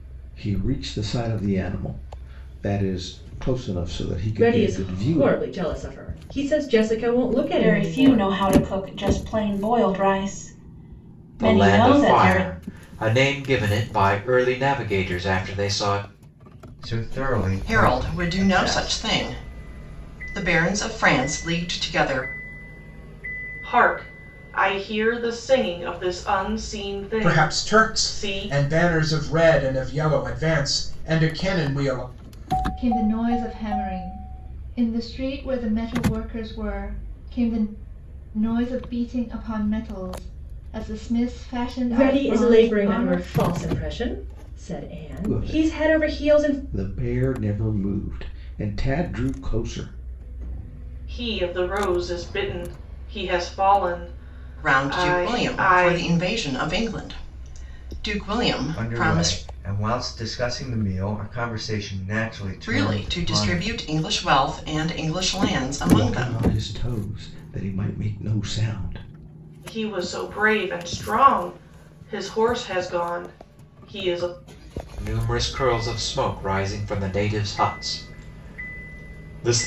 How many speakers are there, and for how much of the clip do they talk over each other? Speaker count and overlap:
nine, about 15%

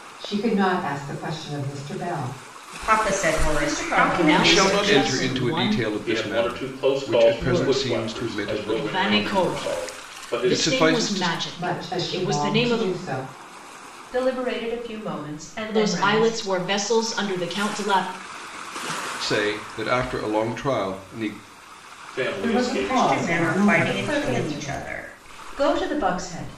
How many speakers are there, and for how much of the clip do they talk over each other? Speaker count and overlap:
six, about 46%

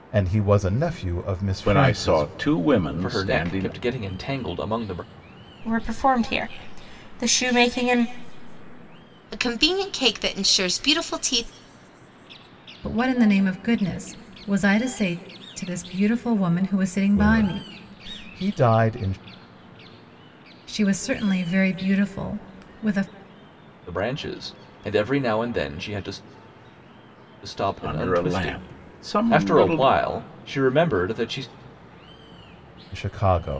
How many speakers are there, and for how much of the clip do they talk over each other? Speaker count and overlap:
six, about 11%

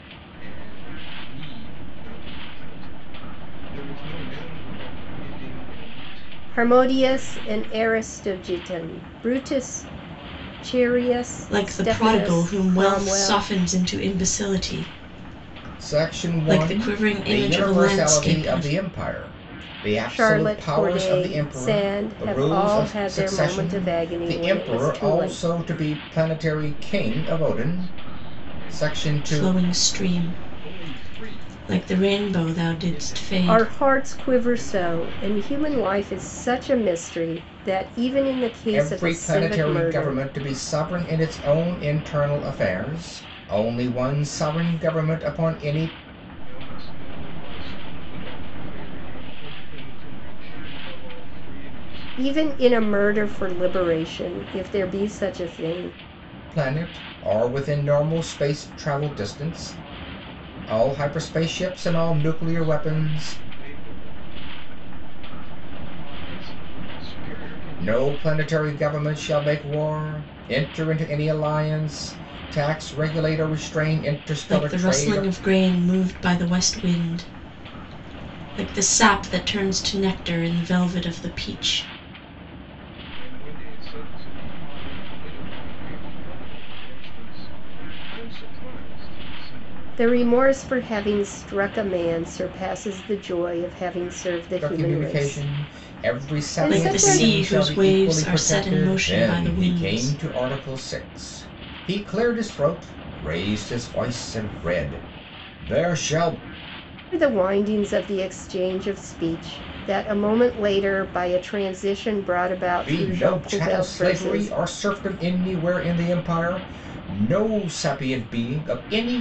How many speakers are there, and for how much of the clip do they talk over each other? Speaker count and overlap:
four, about 28%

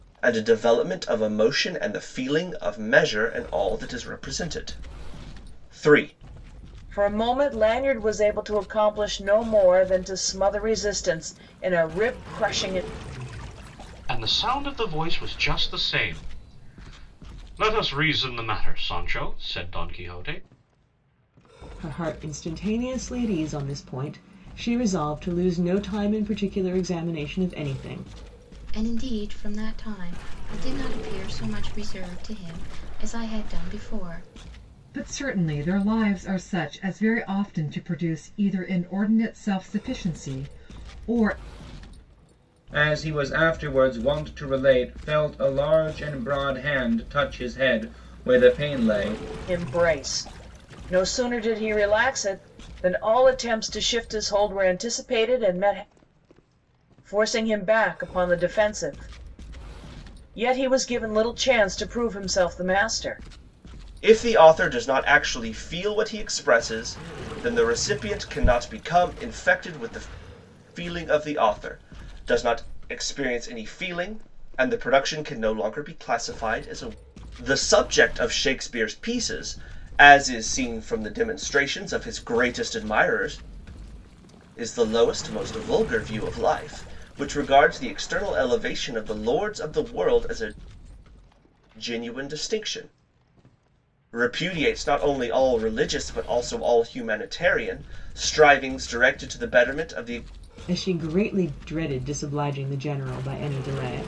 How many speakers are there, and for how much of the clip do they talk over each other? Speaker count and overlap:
seven, no overlap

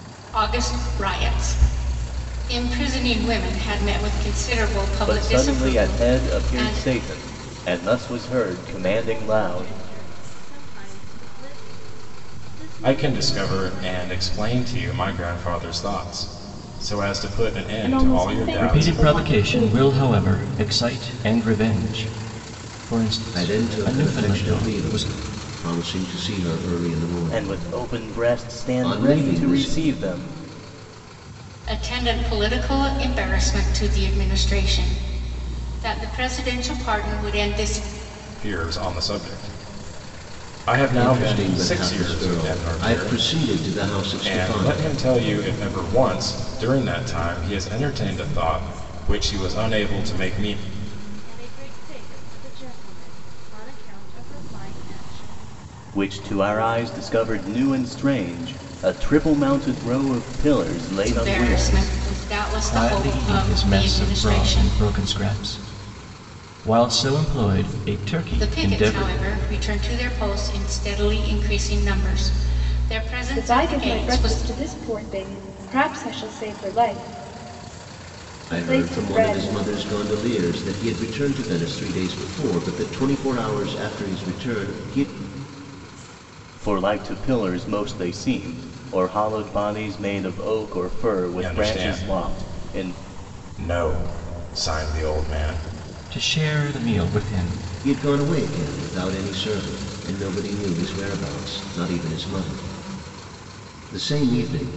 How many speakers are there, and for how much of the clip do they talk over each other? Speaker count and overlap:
seven, about 22%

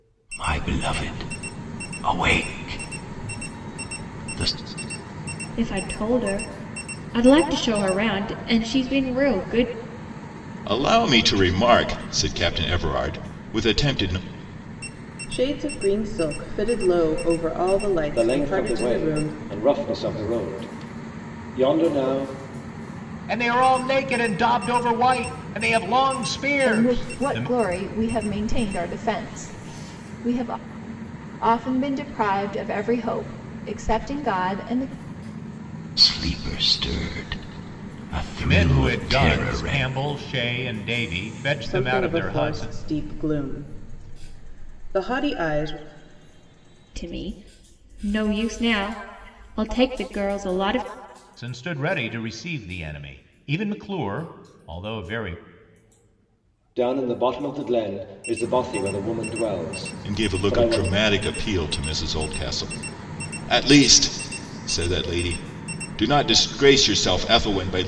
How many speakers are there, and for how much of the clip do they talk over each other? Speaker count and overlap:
seven, about 8%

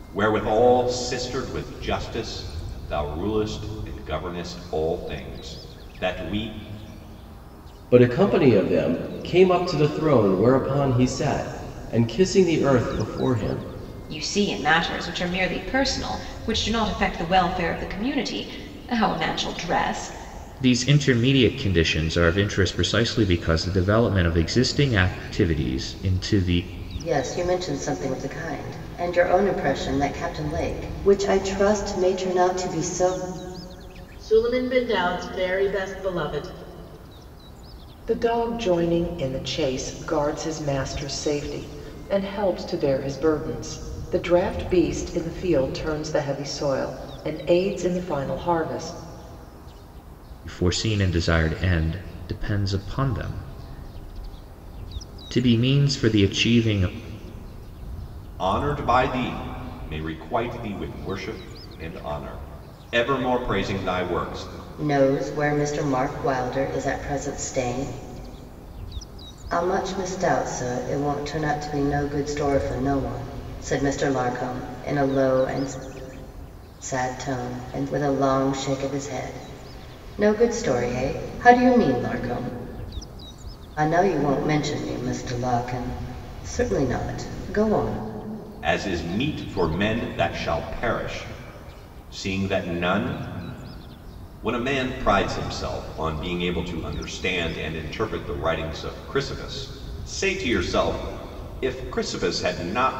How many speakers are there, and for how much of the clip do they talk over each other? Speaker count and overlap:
seven, no overlap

